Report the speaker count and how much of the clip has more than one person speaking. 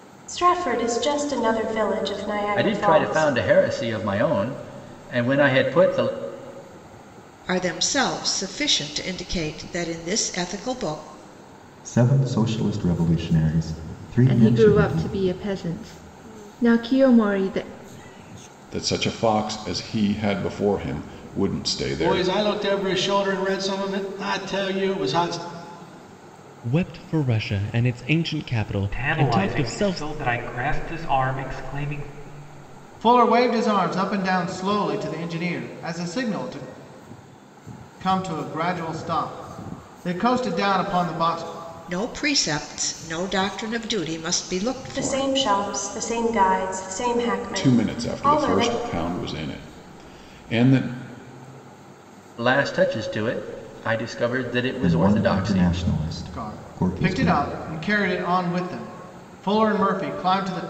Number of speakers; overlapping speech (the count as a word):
ten, about 11%